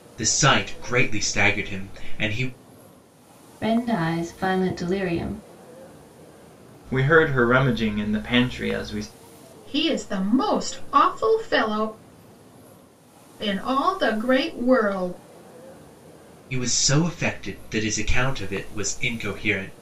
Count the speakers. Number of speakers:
four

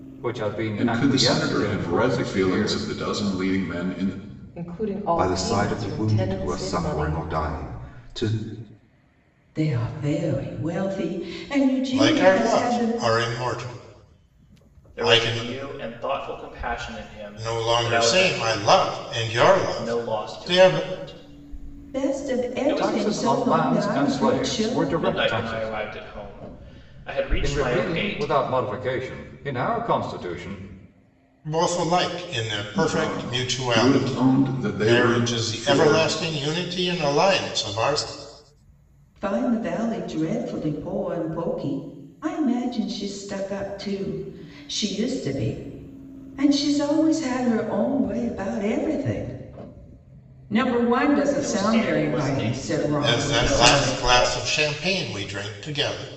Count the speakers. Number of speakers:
seven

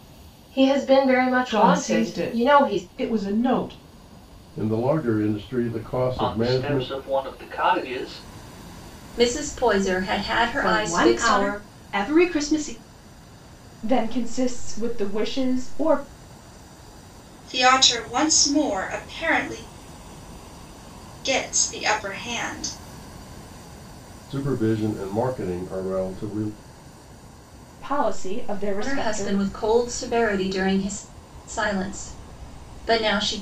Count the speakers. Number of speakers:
eight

